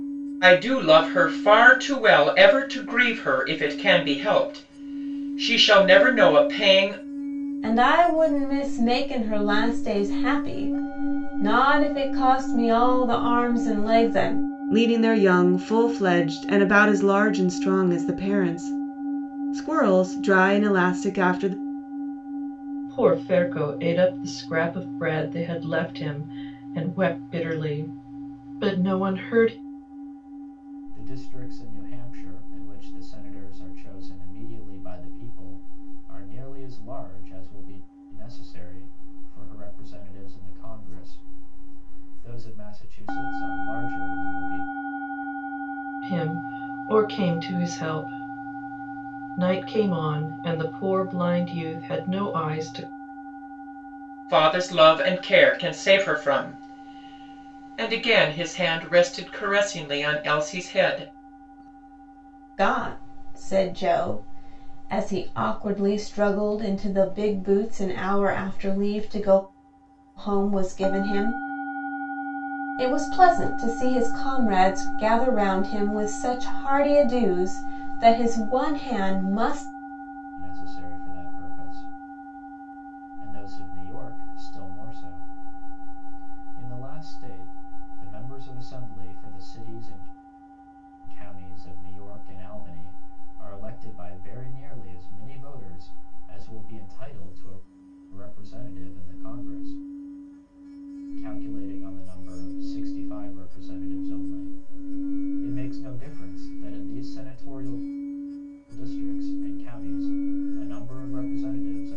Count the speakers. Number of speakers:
5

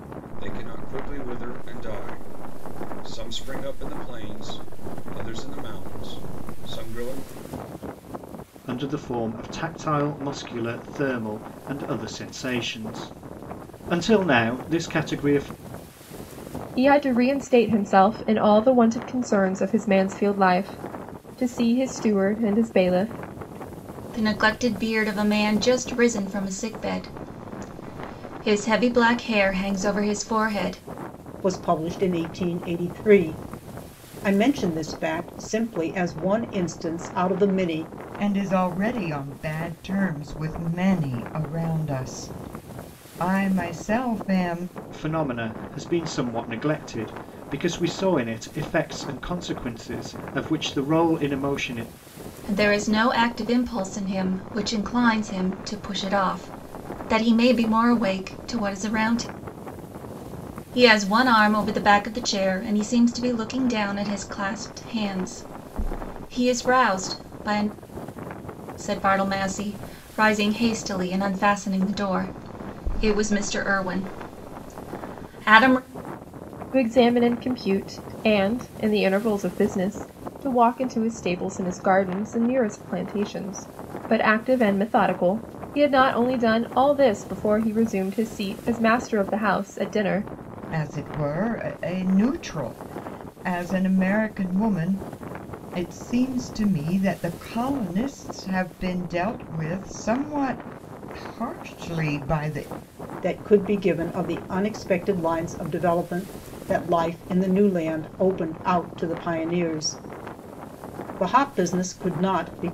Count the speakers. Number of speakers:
6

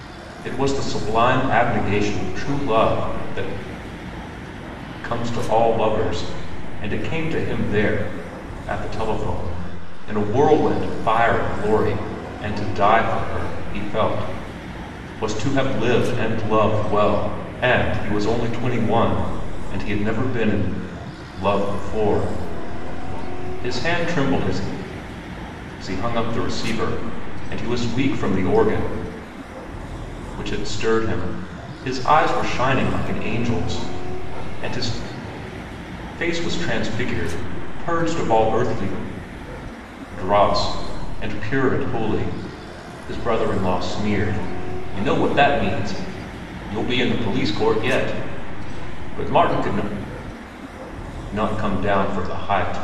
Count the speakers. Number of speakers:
1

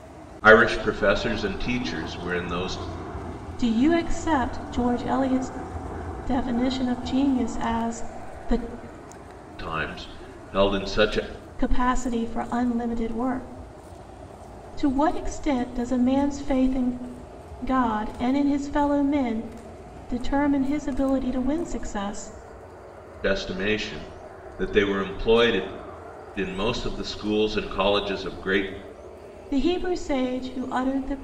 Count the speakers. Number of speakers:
2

